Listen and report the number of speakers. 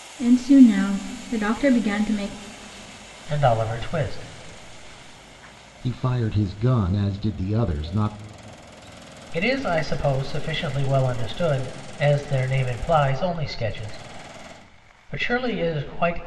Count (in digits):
3